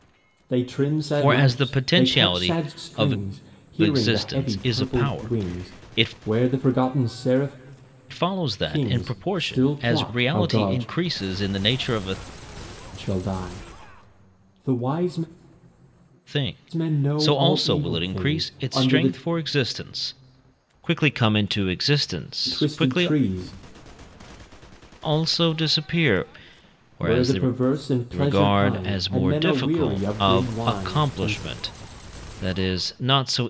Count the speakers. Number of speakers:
2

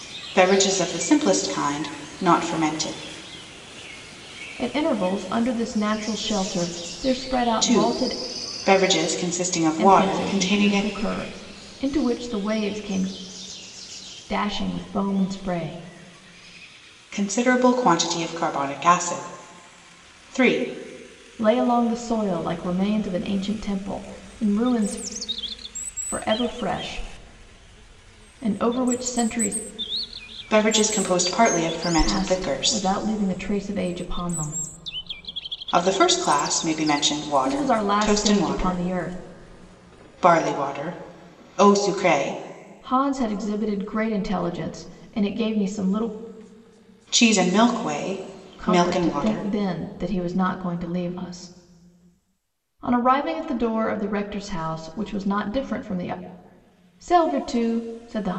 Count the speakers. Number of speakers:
2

